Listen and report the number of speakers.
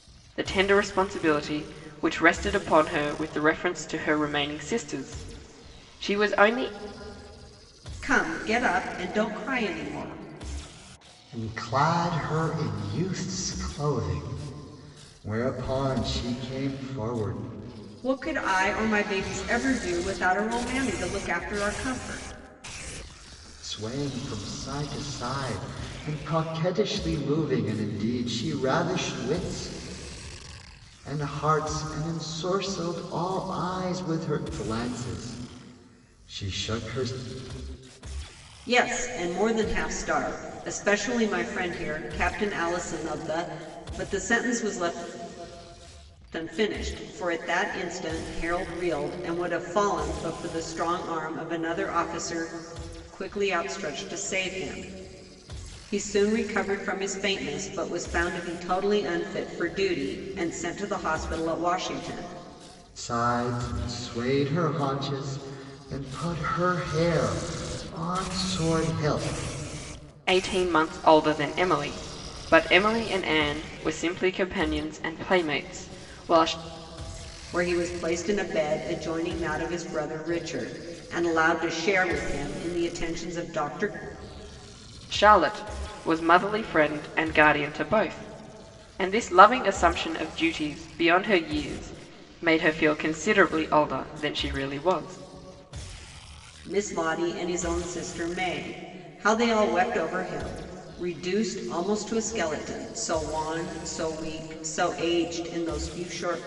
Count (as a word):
three